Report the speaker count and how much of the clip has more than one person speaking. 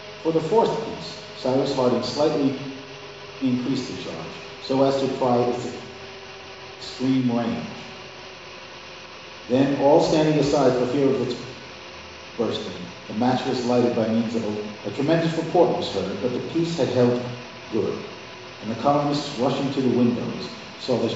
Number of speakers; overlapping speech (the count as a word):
one, no overlap